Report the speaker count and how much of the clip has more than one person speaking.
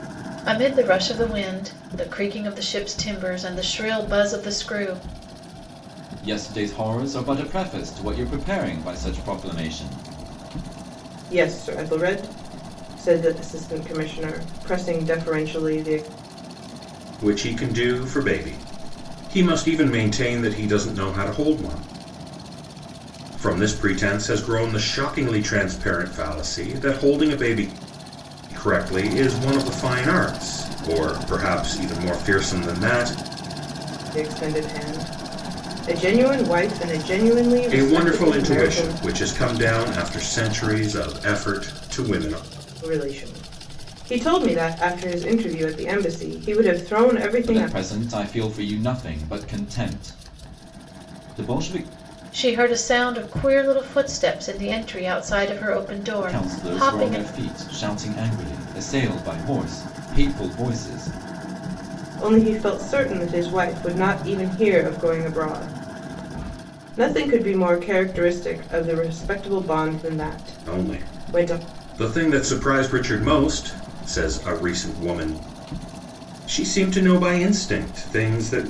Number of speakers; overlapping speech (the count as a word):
four, about 4%